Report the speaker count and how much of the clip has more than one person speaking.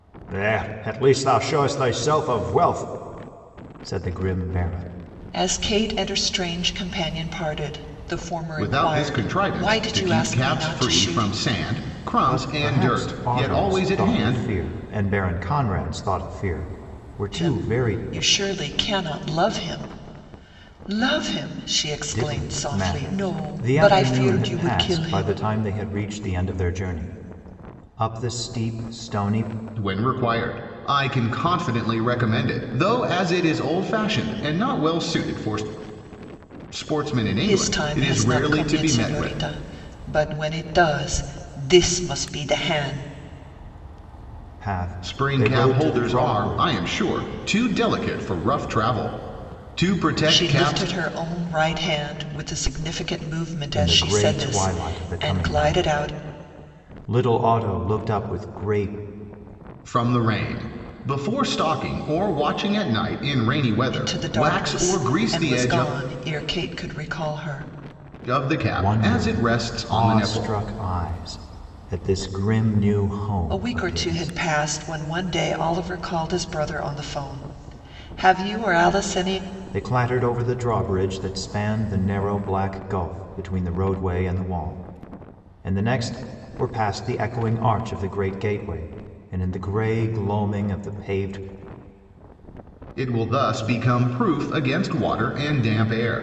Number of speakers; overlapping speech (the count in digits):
3, about 21%